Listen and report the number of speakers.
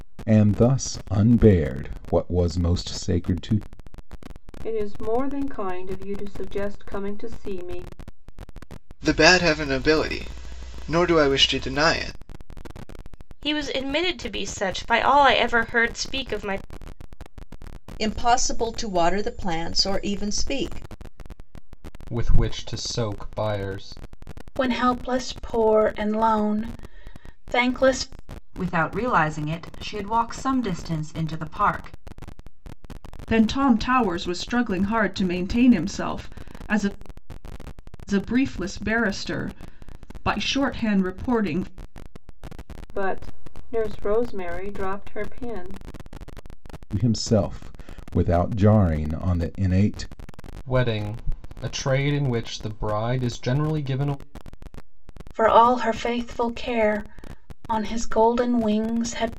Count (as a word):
nine